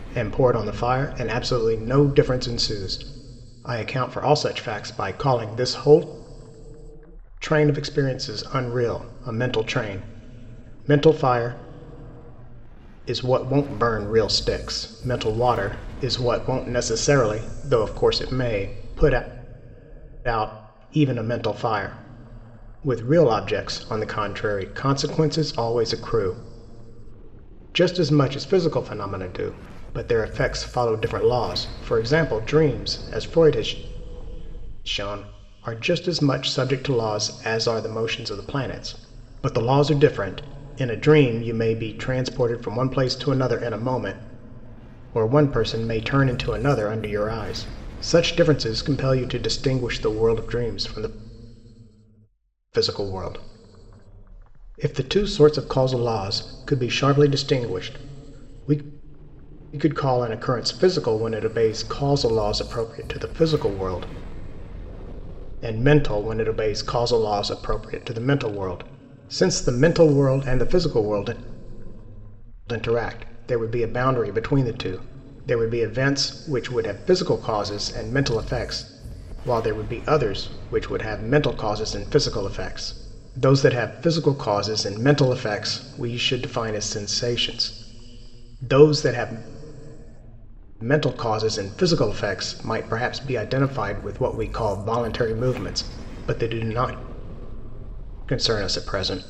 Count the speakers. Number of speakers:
1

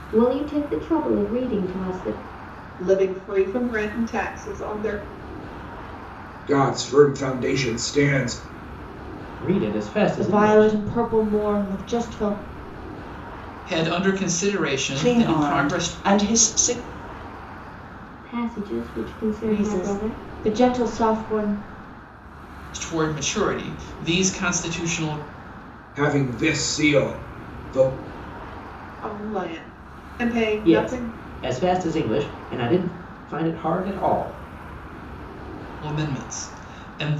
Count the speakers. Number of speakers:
7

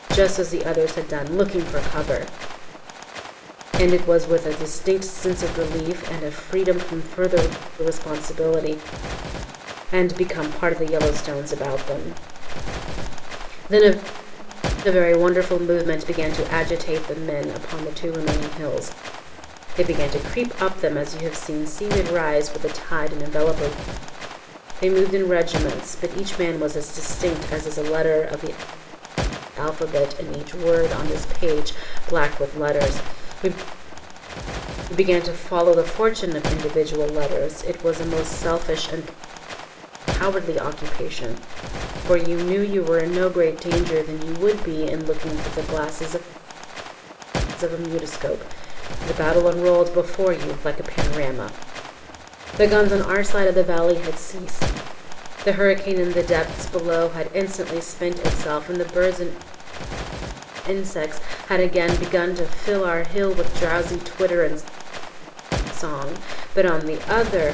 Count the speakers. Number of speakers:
1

